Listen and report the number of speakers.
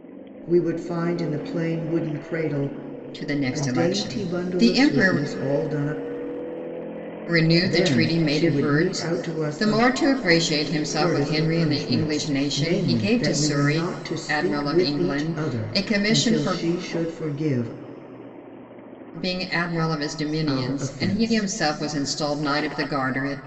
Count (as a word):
two